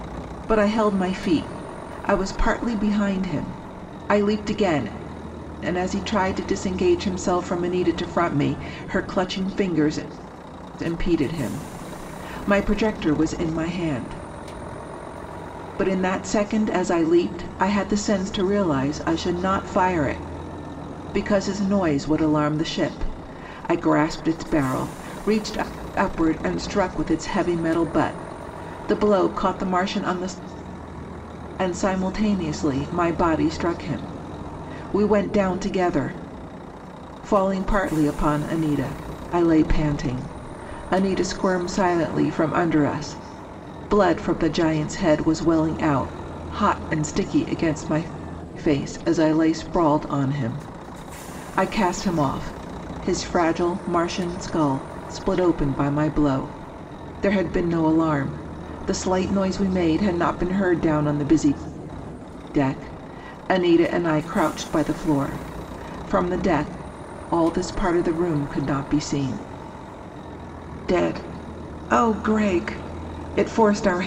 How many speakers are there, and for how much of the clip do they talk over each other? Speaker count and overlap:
1, no overlap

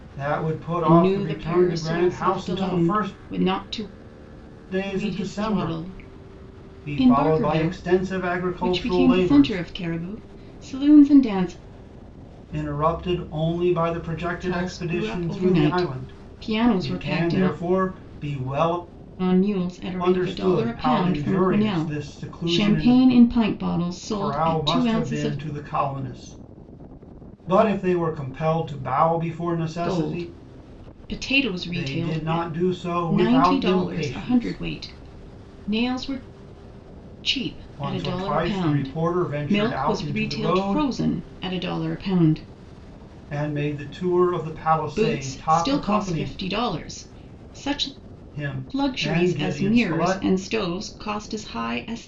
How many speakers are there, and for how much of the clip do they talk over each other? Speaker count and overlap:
2, about 41%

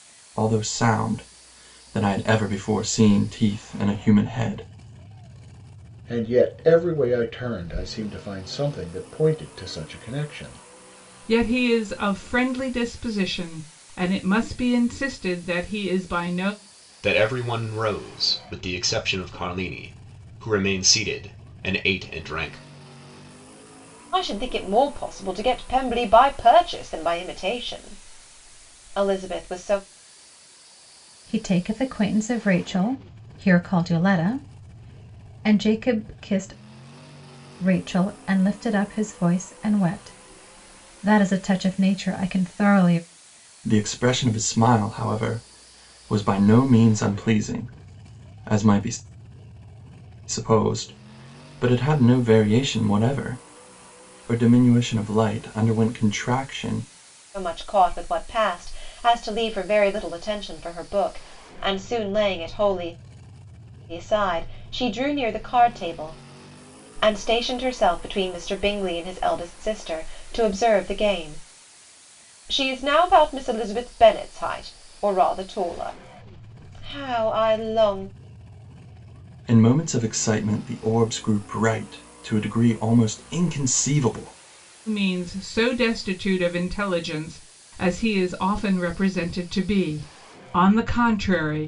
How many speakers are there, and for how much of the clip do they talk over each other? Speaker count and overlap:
6, no overlap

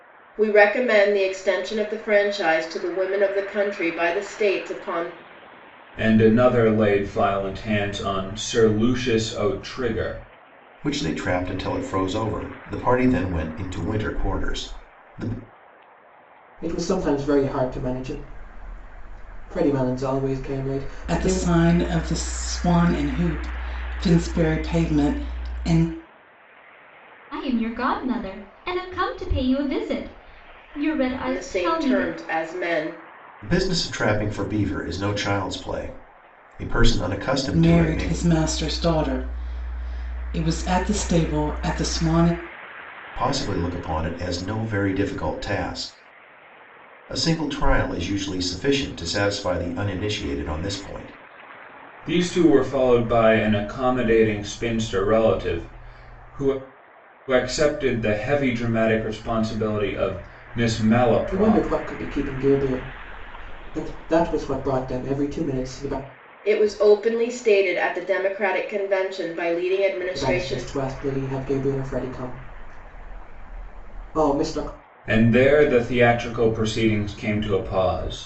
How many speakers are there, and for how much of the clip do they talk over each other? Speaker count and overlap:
6, about 4%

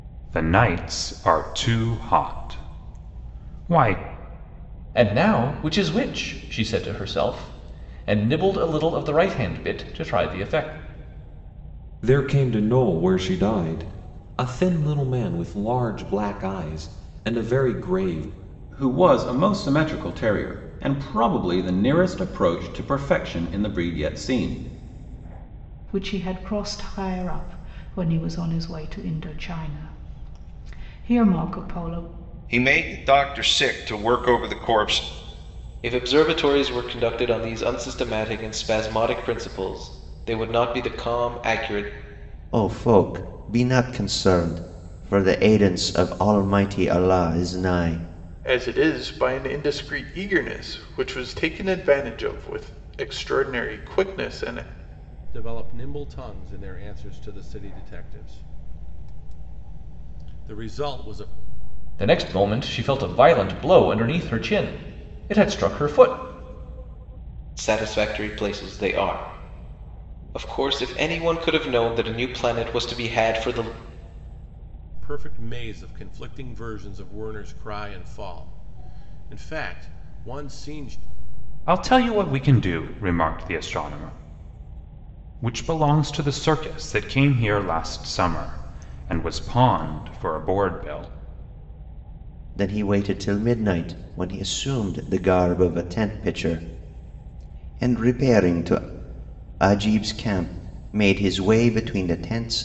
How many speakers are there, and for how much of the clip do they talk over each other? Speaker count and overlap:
10, no overlap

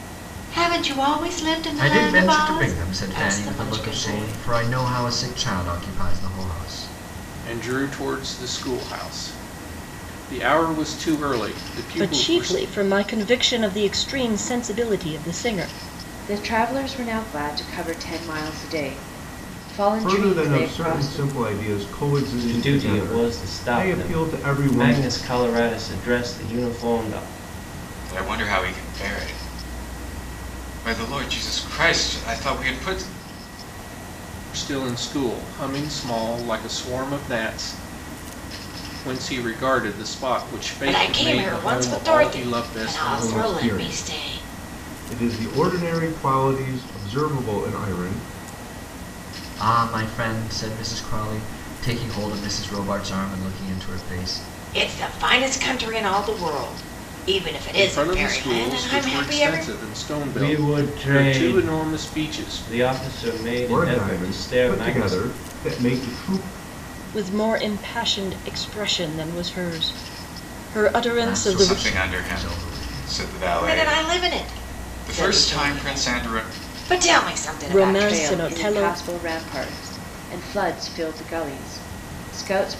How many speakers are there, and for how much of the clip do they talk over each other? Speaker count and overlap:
8, about 28%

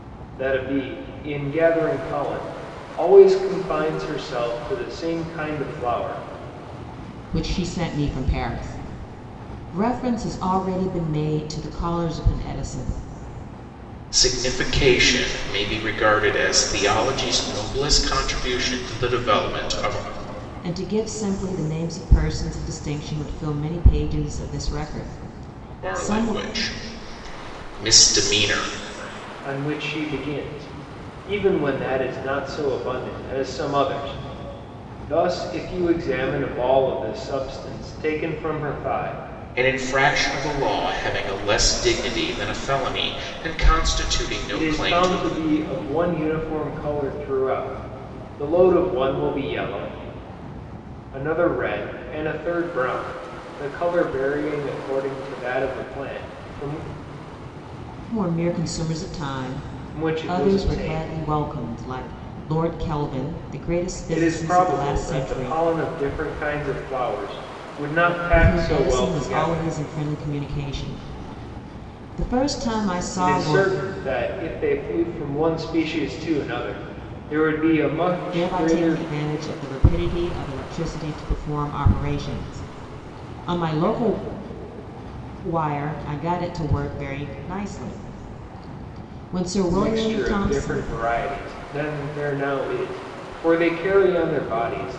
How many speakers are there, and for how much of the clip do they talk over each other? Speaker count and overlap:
3, about 8%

